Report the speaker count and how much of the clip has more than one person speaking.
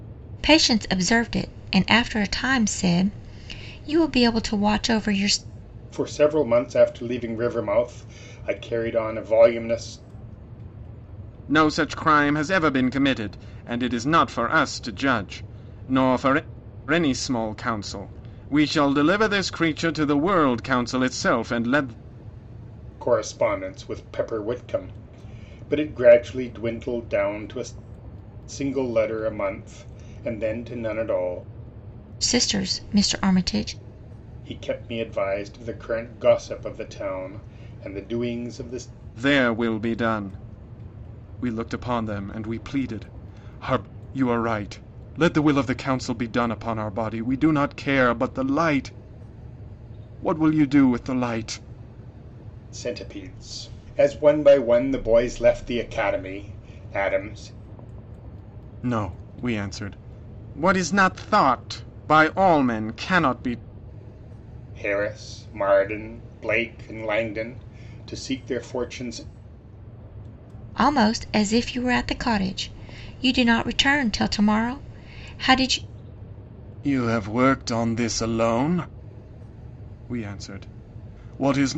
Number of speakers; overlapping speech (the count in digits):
3, no overlap